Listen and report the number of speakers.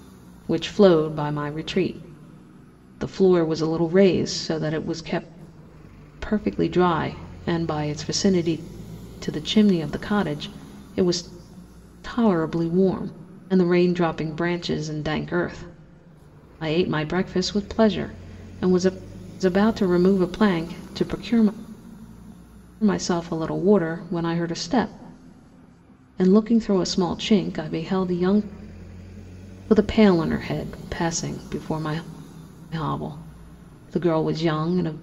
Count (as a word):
one